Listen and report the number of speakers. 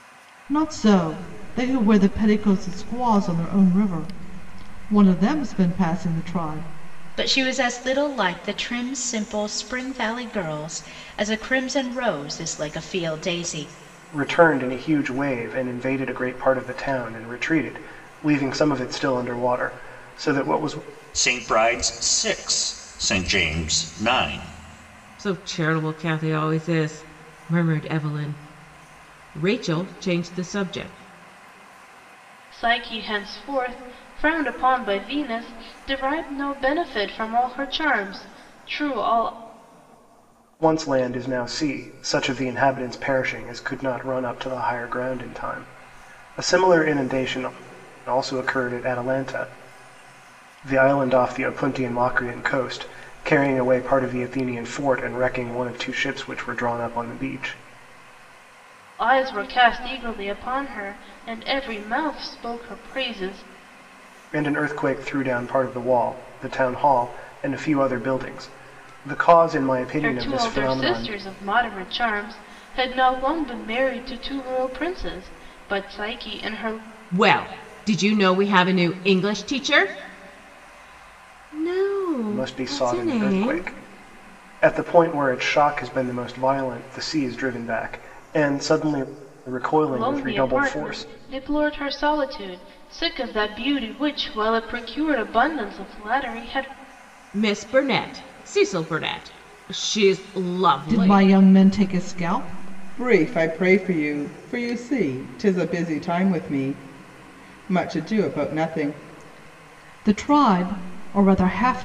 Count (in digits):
6